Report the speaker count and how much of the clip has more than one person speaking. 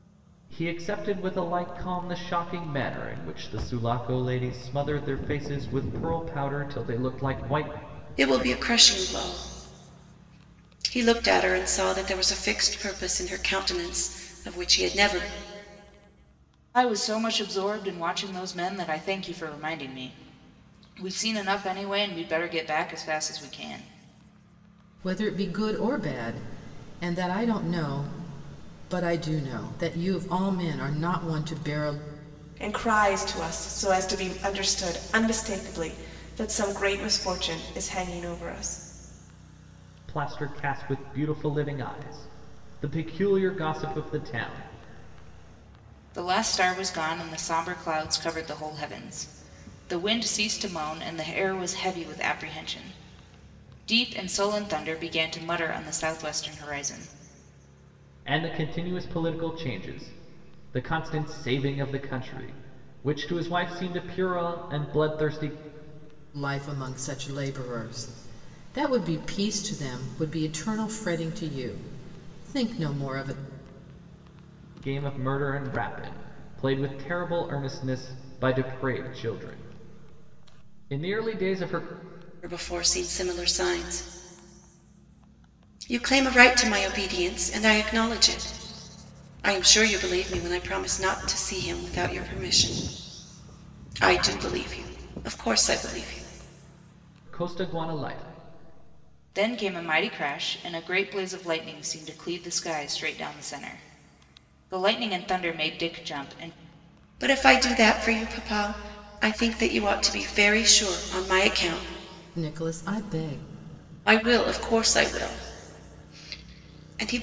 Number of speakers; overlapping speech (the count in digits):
5, no overlap